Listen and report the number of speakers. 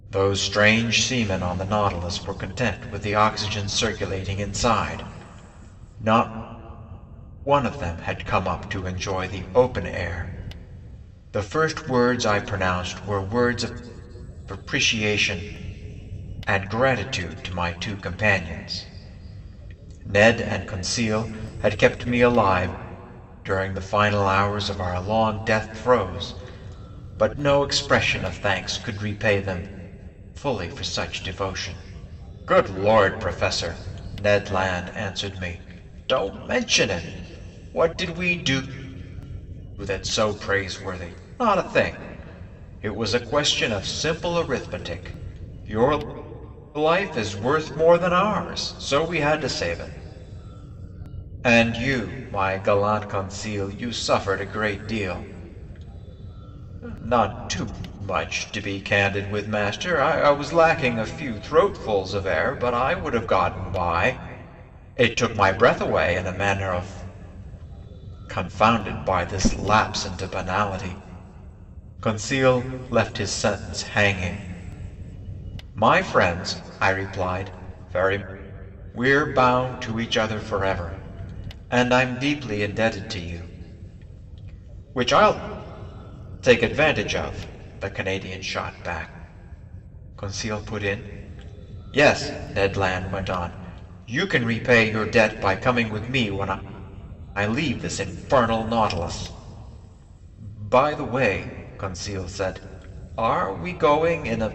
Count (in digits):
1